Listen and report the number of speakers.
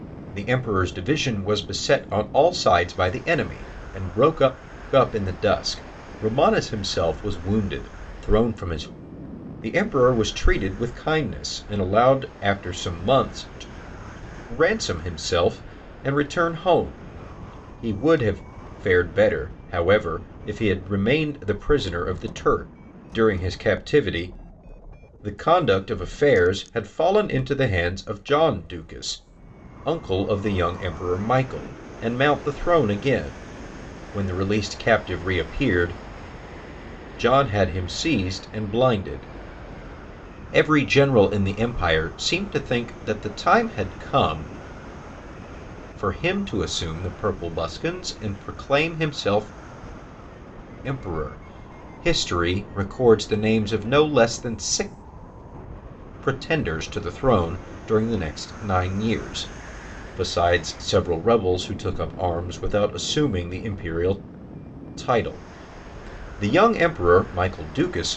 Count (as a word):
one